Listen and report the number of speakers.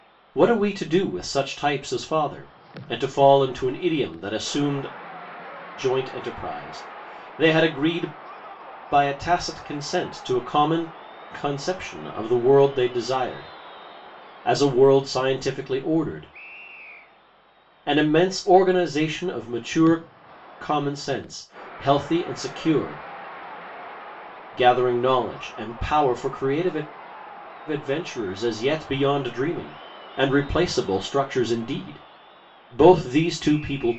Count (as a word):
one